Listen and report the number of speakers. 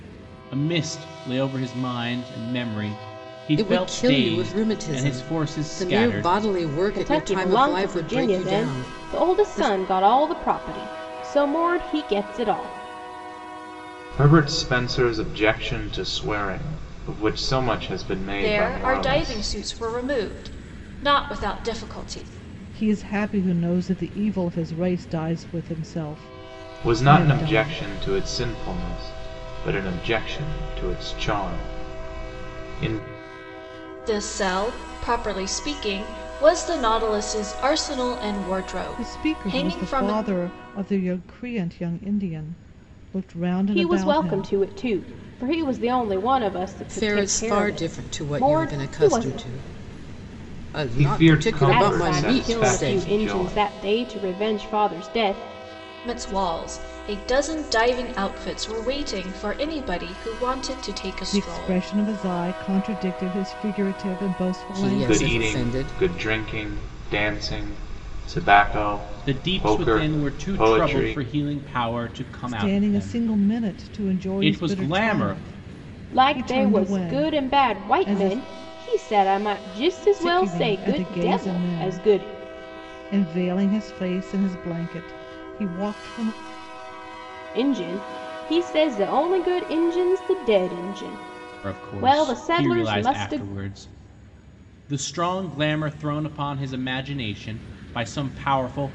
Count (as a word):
six